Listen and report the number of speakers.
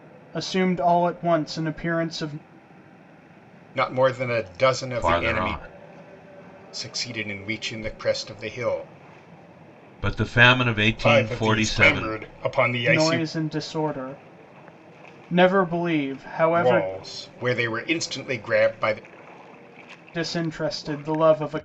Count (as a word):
three